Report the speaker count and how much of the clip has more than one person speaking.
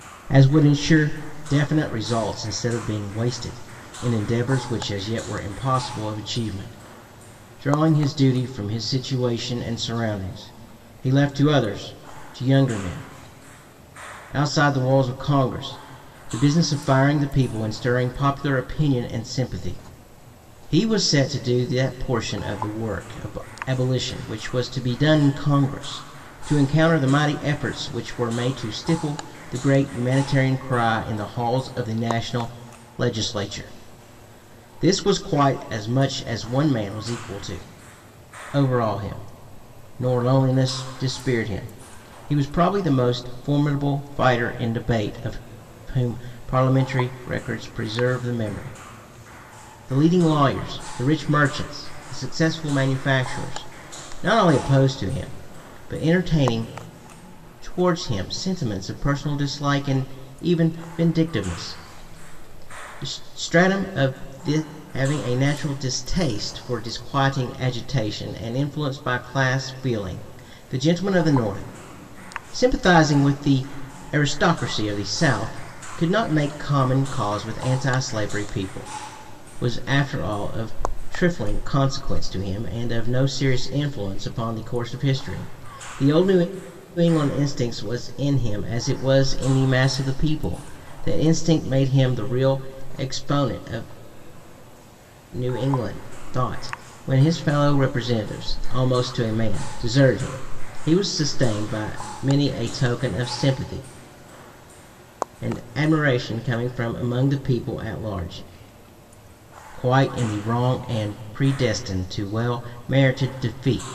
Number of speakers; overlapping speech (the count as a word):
one, no overlap